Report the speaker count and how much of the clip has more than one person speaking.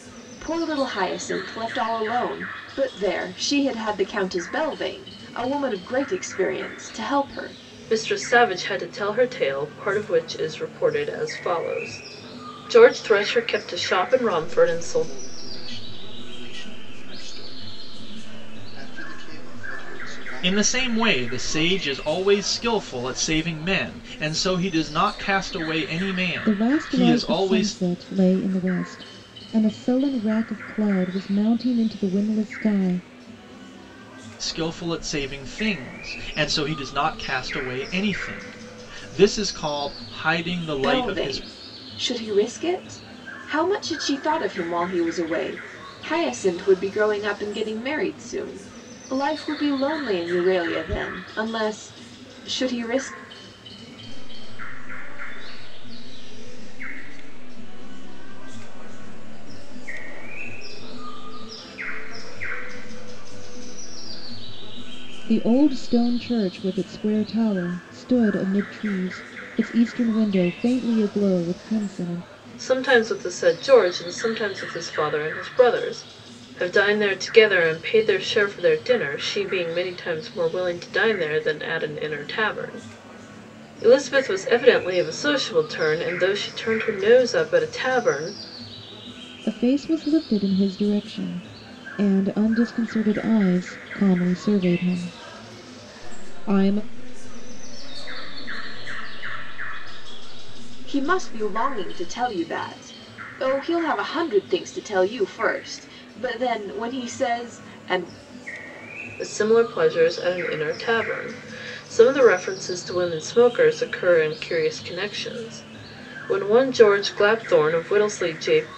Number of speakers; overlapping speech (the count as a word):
five, about 6%